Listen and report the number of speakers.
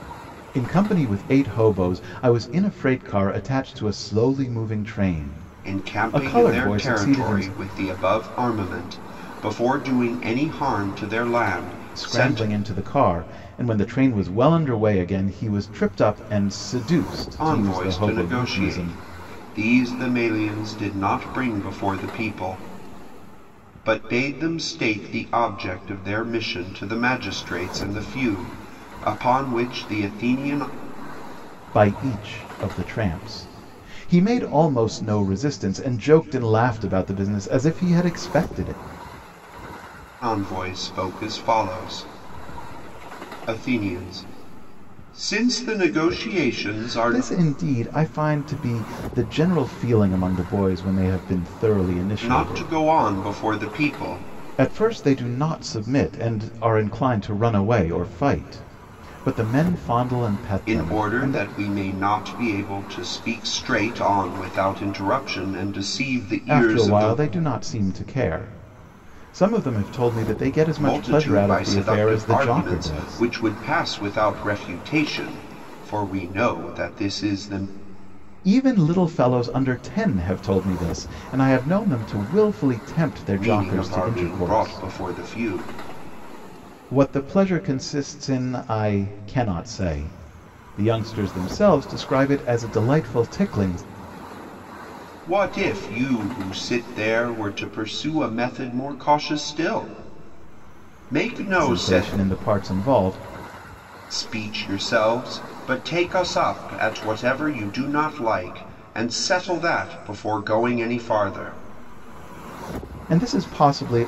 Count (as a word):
two